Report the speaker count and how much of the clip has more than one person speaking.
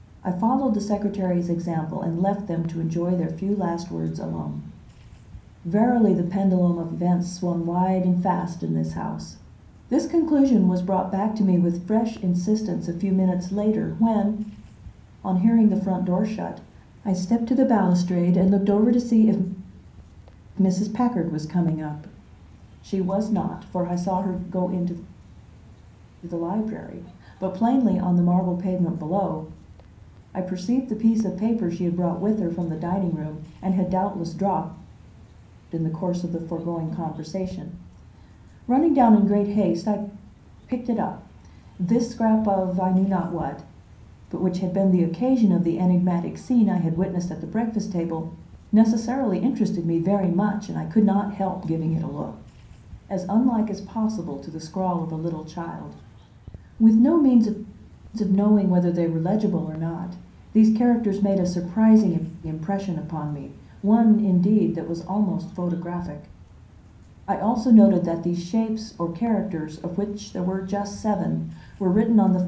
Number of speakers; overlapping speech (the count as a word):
one, no overlap